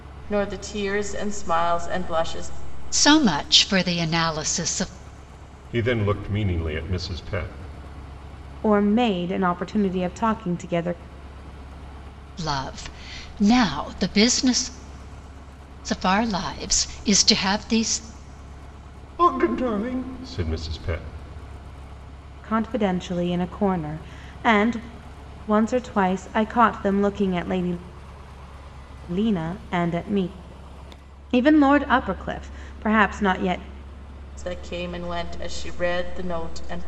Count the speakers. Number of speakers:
four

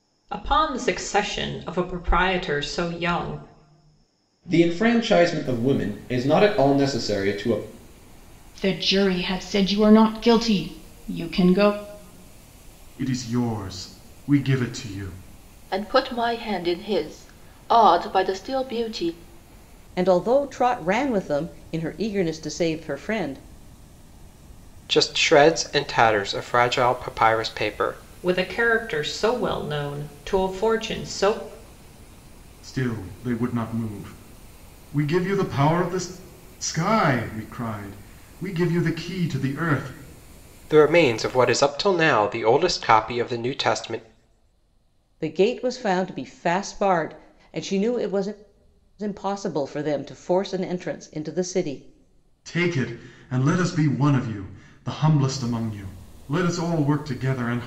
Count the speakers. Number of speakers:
seven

